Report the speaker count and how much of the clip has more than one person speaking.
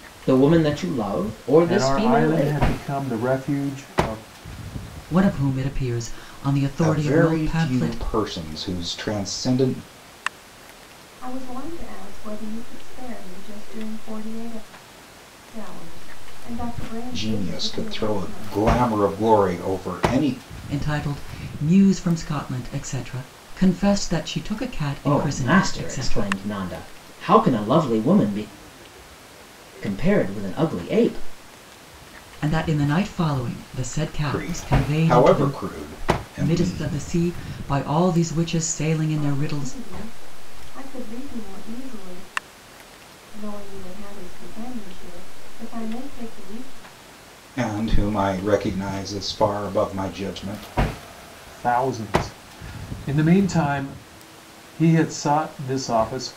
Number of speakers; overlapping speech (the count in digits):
5, about 14%